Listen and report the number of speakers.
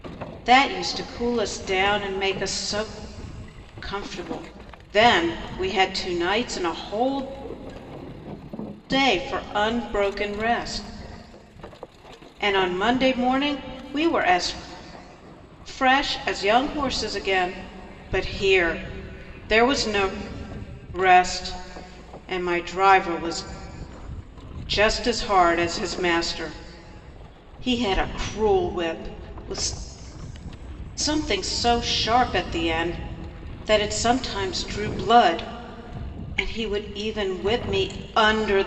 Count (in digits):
1